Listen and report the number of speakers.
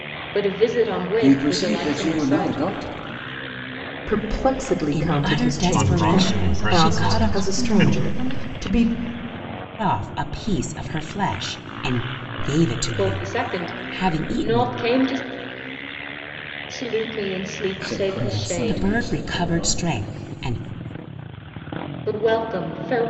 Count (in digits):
6